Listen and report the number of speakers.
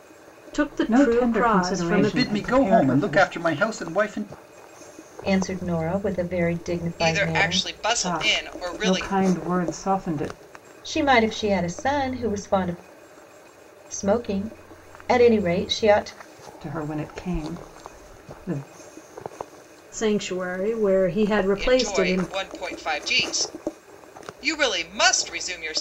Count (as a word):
five